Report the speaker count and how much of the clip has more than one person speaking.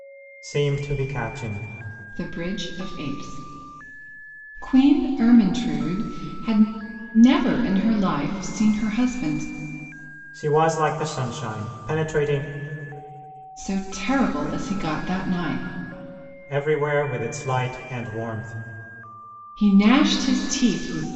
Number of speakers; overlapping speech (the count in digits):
2, no overlap